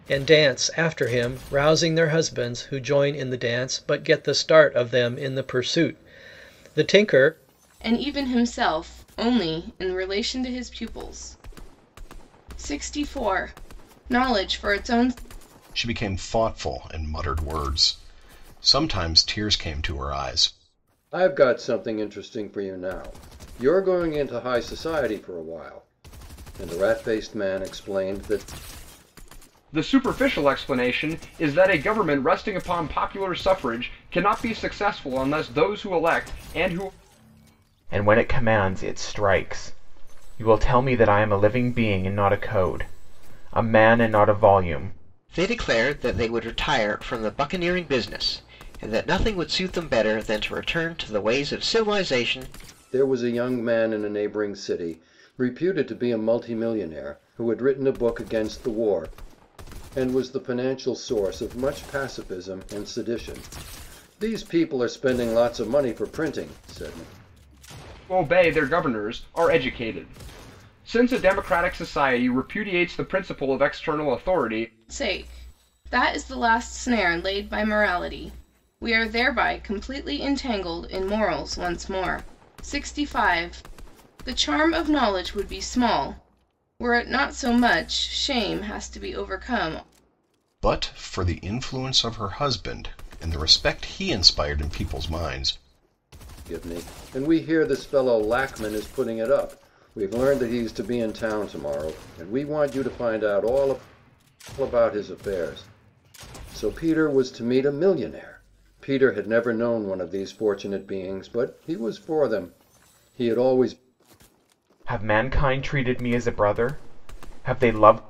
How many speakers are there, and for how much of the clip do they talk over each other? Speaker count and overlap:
7, no overlap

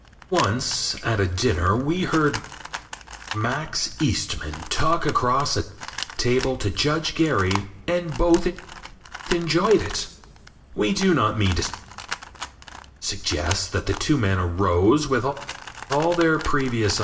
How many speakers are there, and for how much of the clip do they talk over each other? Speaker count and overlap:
1, no overlap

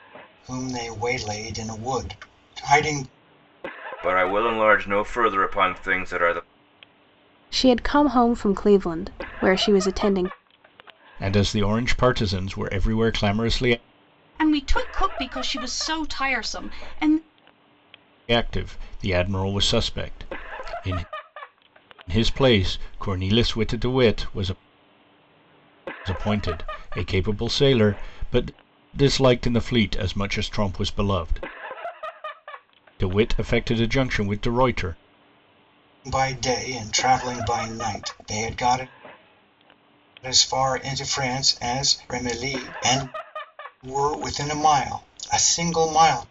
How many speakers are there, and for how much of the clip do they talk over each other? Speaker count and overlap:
5, no overlap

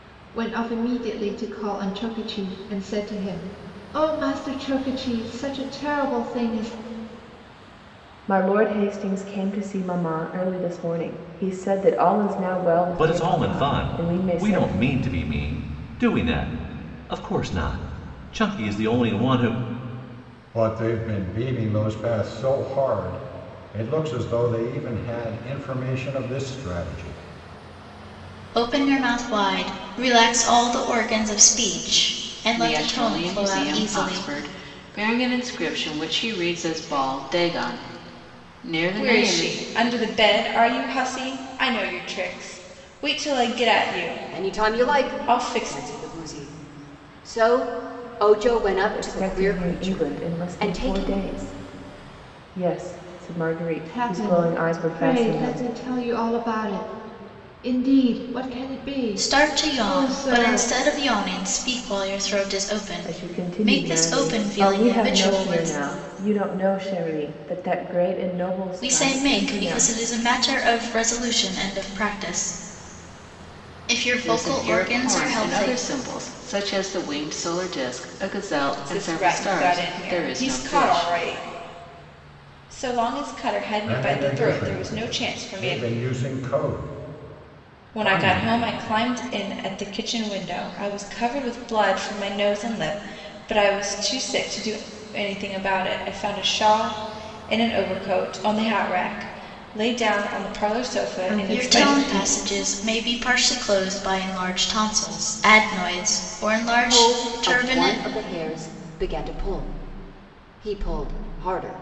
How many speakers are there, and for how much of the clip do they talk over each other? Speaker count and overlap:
8, about 21%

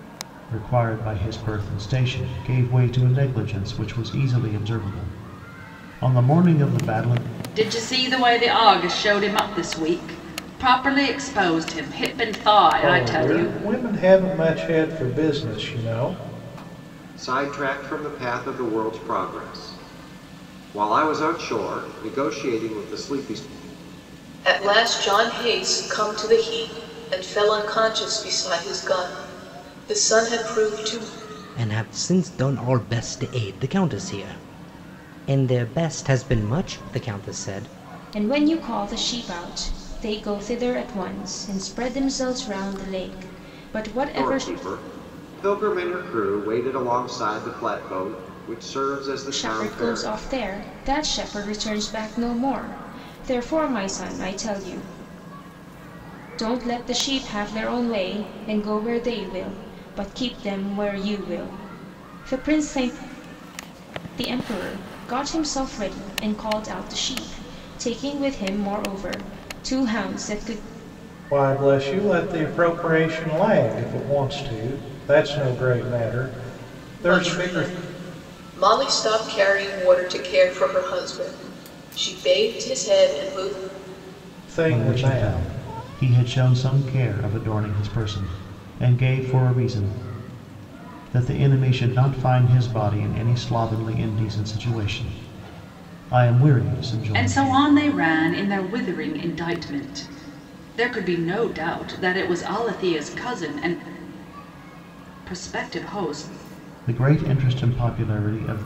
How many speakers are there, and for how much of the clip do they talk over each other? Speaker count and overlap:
7, about 4%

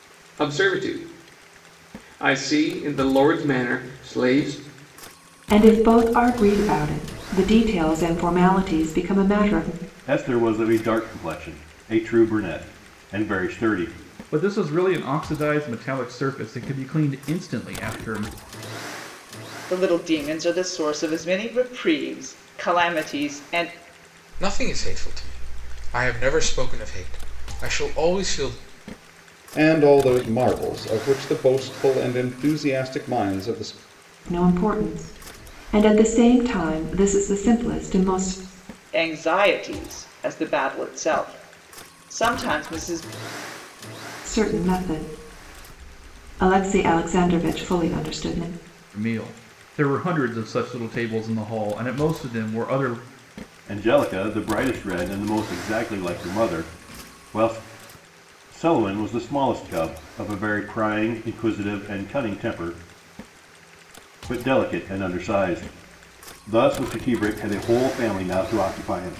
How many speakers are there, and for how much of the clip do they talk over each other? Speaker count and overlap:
7, no overlap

